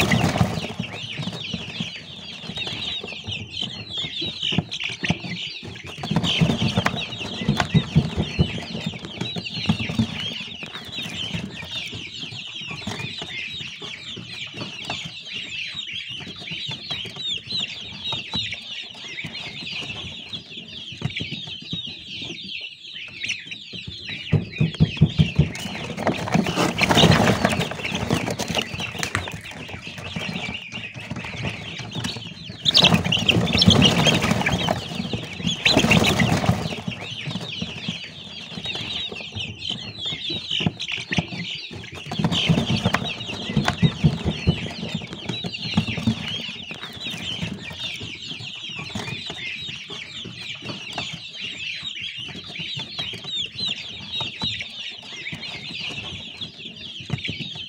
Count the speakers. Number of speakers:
zero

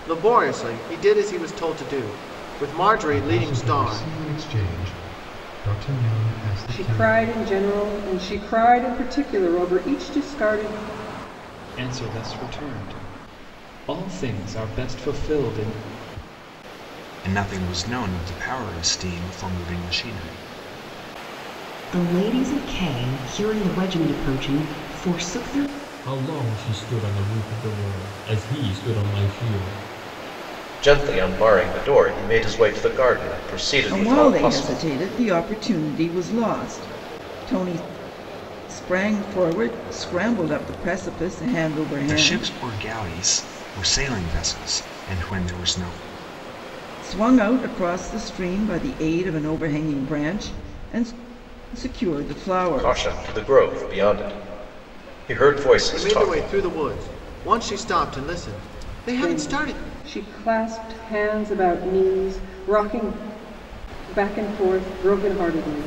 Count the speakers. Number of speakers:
nine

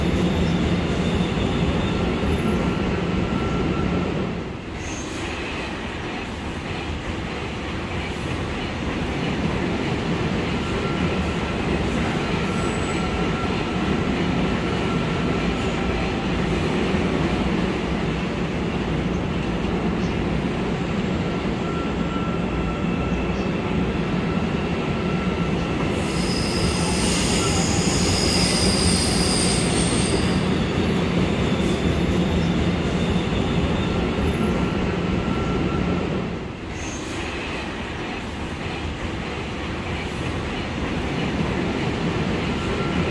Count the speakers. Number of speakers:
zero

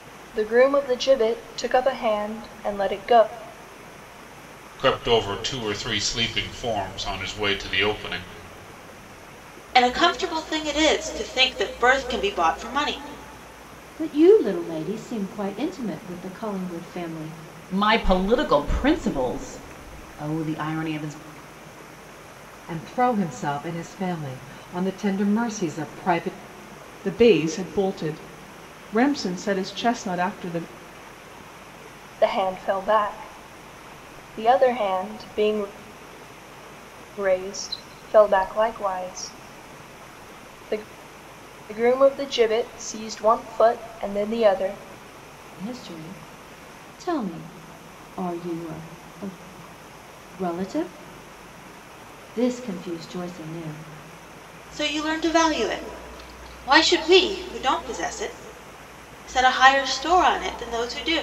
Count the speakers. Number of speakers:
seven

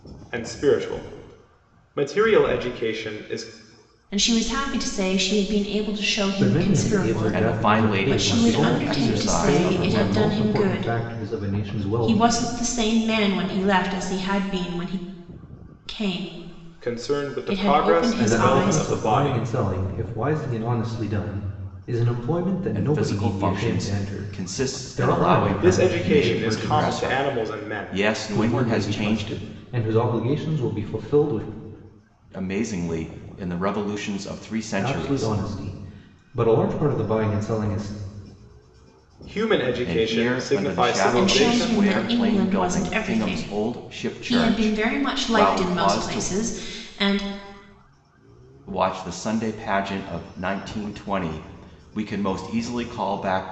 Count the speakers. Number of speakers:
four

